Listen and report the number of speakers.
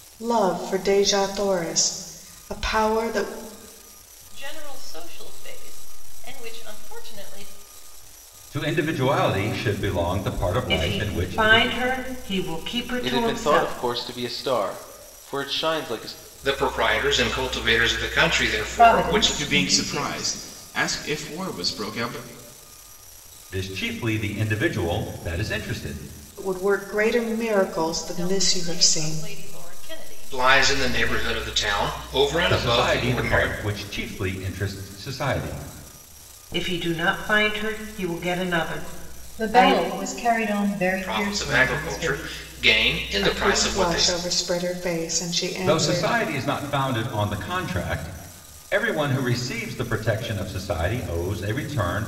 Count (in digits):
8